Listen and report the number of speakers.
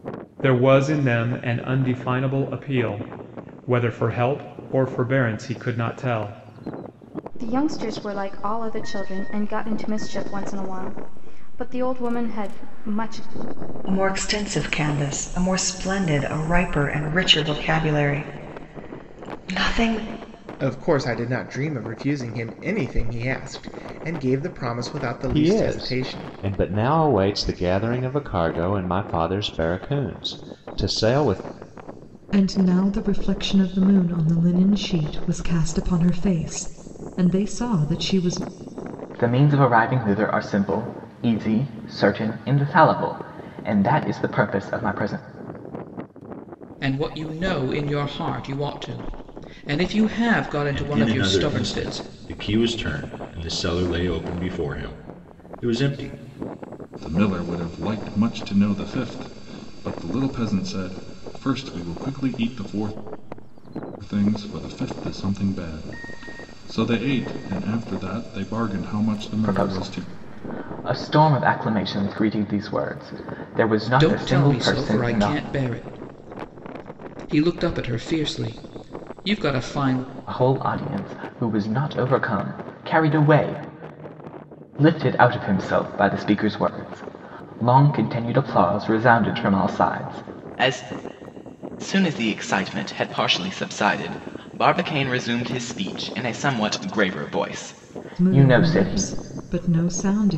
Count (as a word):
ten